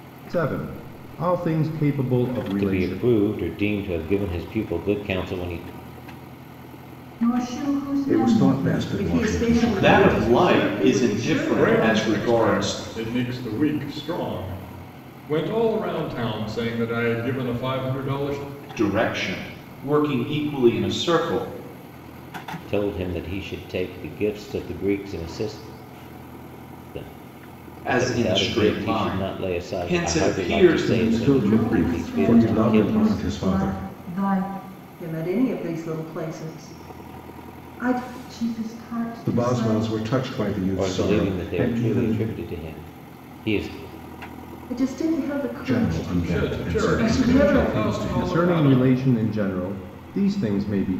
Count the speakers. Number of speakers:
seven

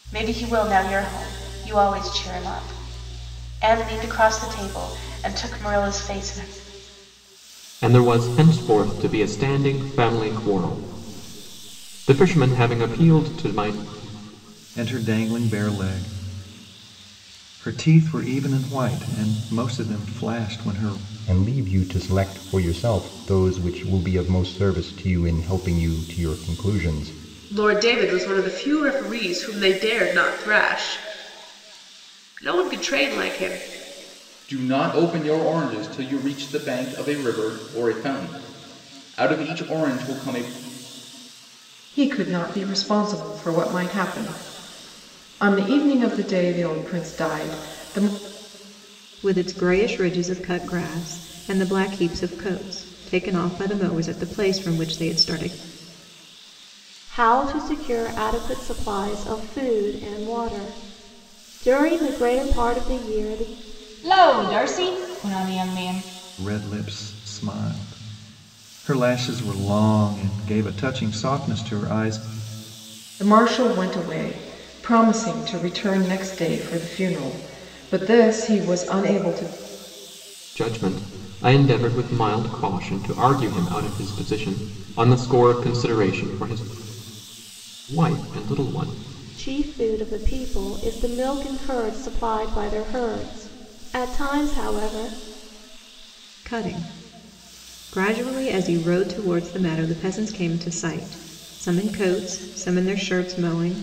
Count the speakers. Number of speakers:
ten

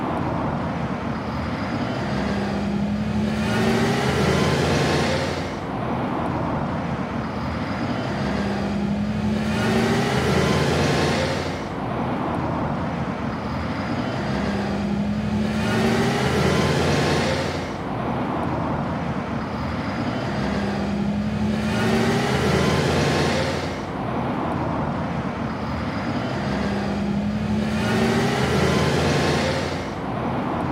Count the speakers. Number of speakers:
zero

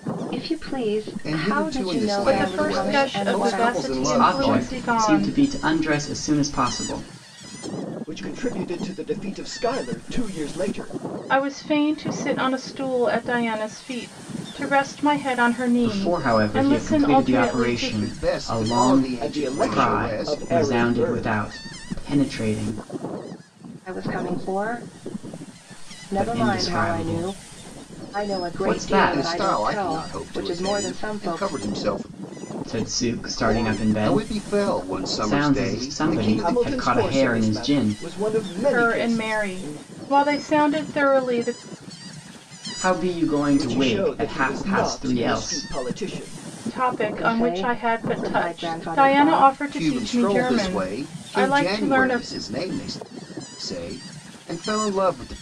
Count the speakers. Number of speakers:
five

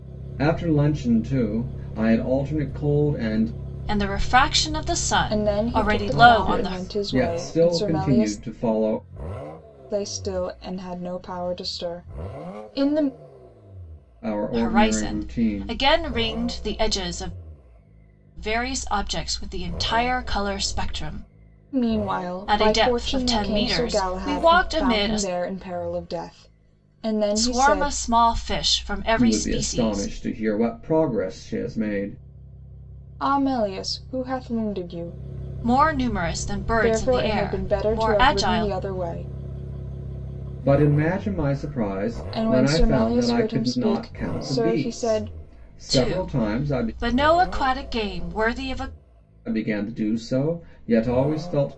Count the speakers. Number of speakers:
three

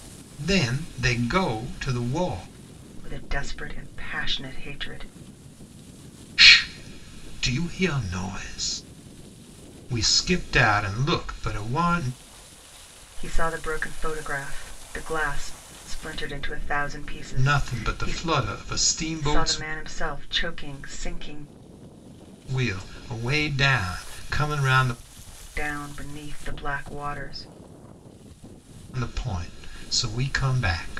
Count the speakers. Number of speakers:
two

